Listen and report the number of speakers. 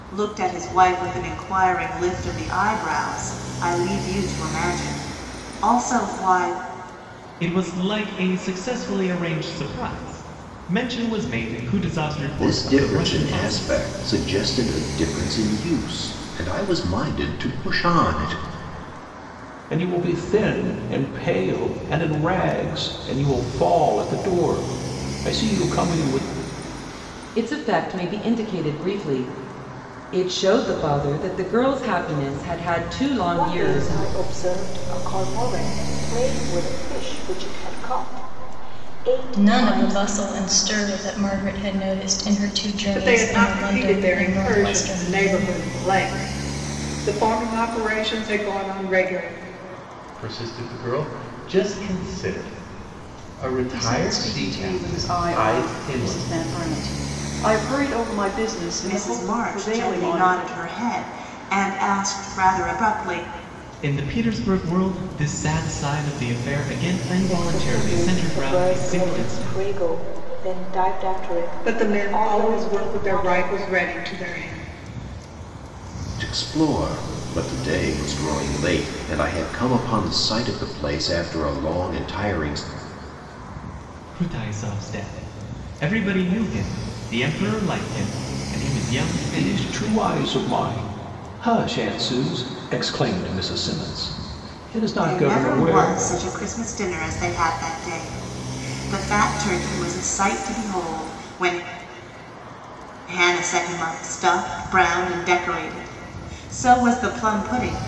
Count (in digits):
10